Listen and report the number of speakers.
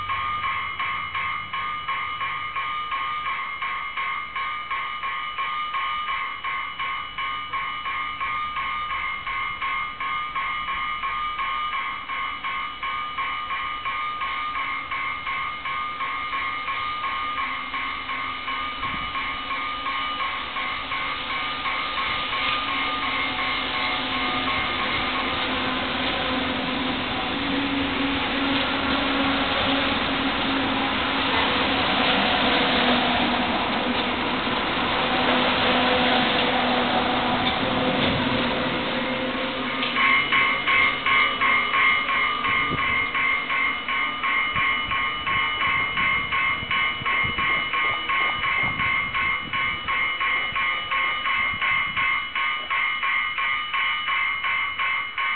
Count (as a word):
zero